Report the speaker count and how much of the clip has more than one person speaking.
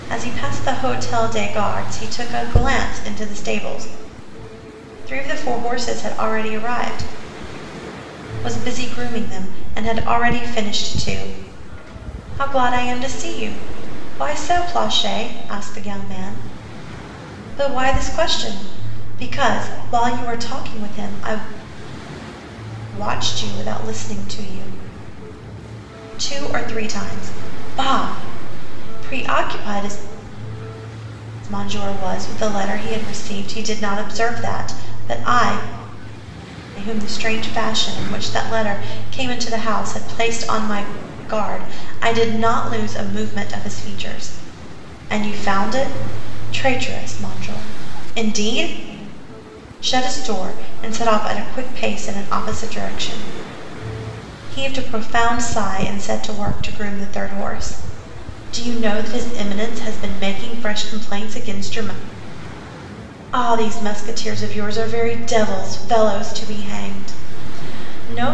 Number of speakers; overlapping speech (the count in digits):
1, no overlap